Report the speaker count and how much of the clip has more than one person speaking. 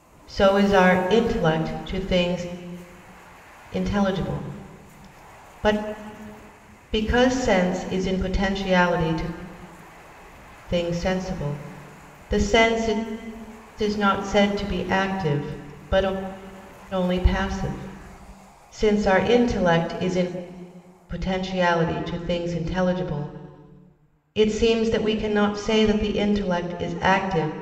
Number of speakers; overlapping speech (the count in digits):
1, no overlap